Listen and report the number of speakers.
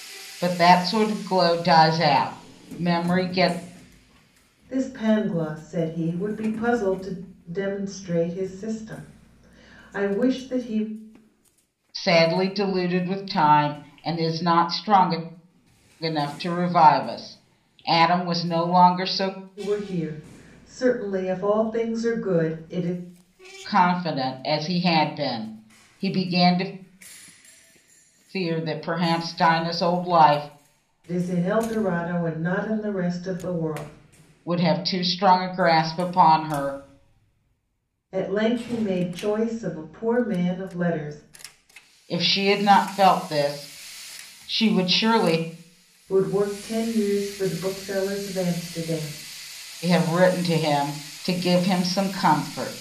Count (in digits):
2